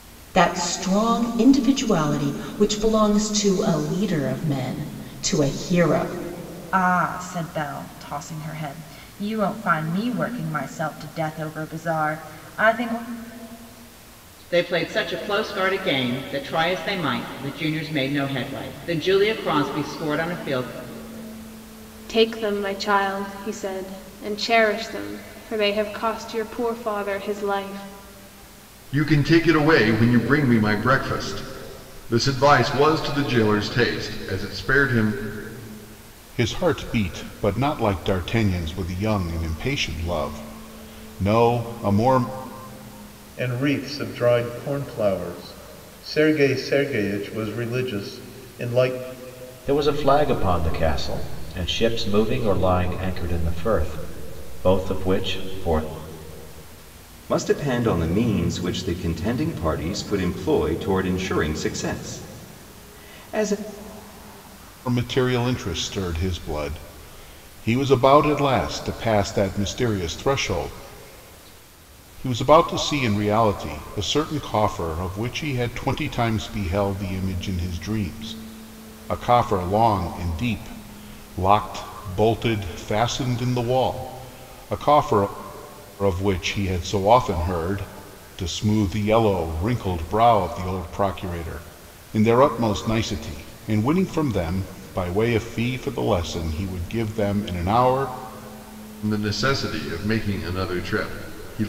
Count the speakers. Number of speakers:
nine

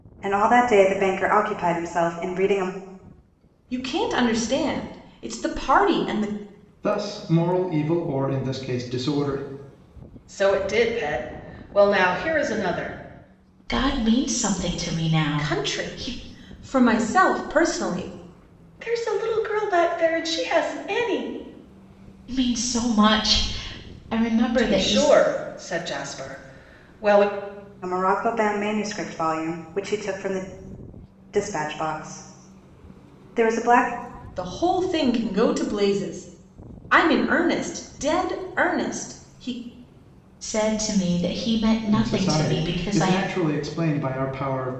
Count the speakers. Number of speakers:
five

